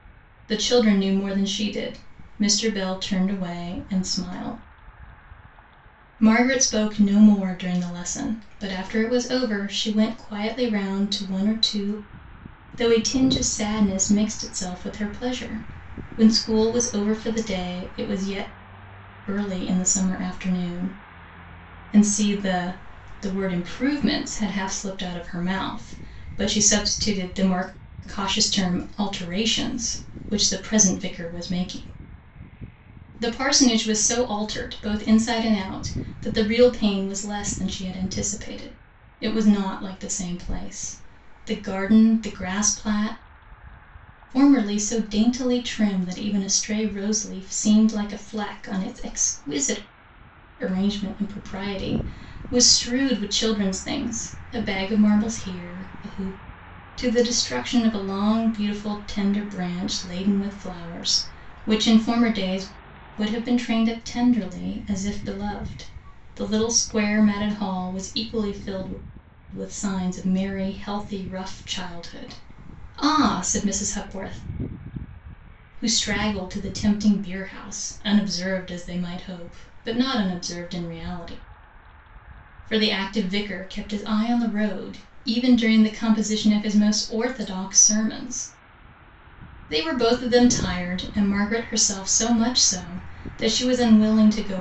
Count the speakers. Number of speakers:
one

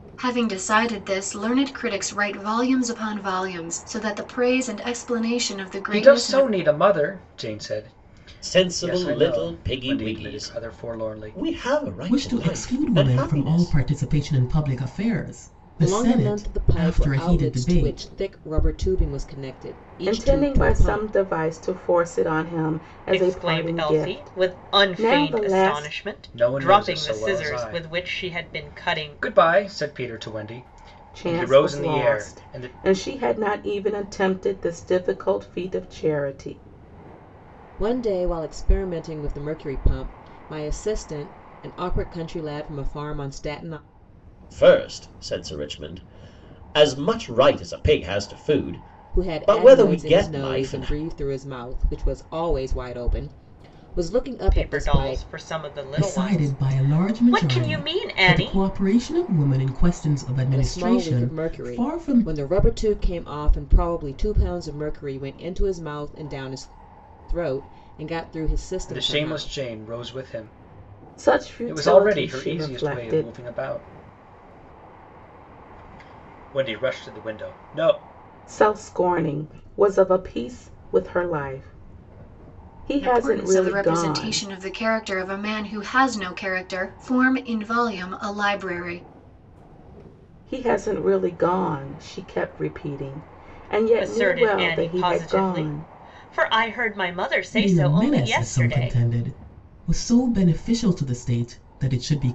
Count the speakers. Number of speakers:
seven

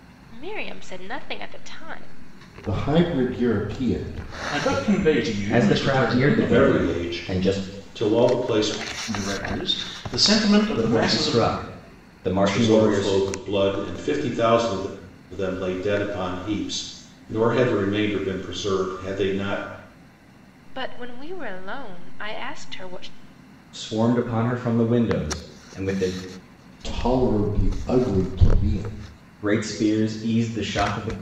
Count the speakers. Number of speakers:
five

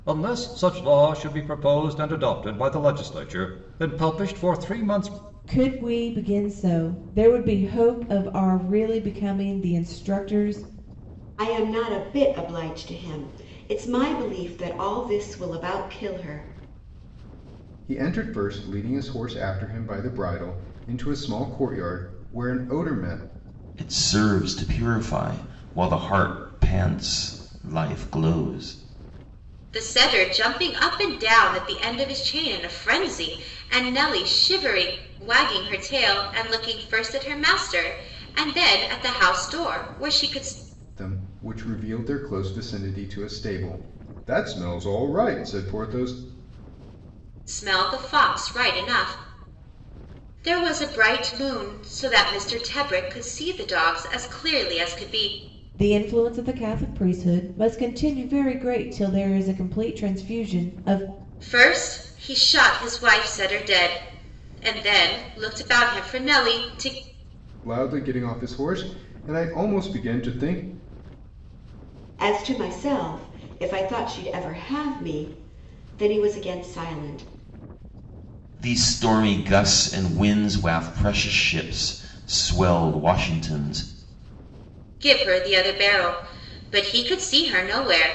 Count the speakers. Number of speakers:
six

